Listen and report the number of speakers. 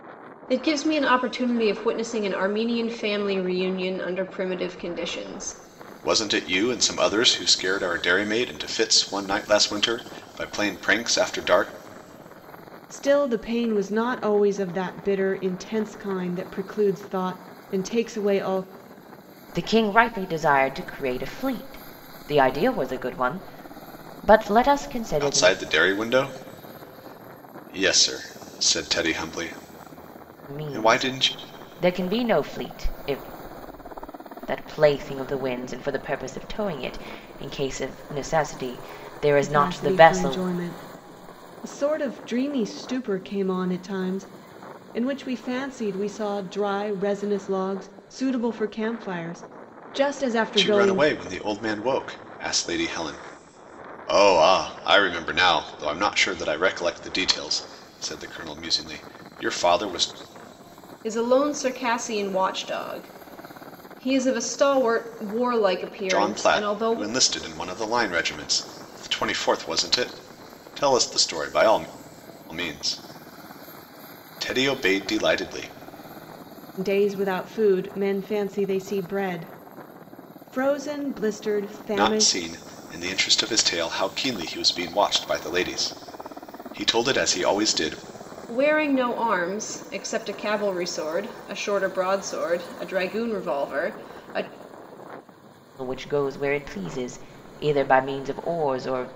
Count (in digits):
4